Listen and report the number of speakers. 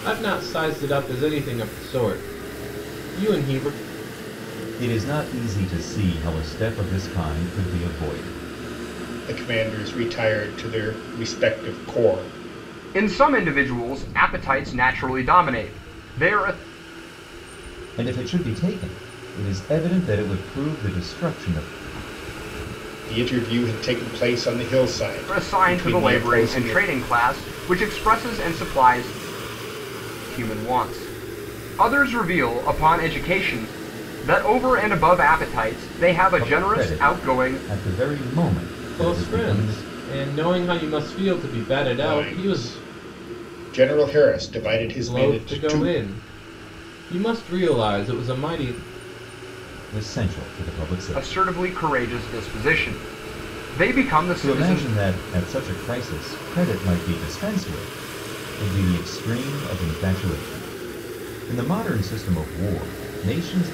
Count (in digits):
4